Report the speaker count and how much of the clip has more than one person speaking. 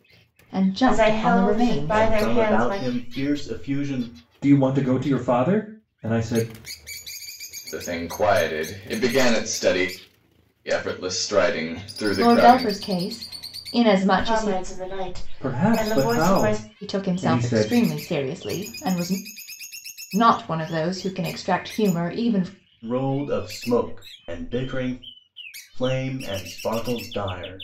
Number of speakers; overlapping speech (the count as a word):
five, about 19%